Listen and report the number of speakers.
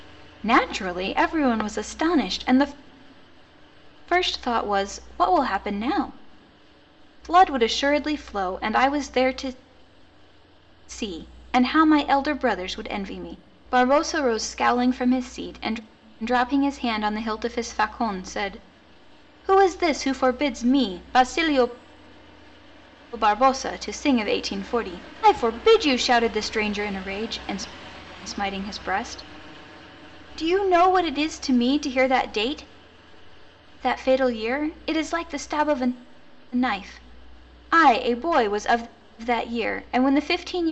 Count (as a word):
one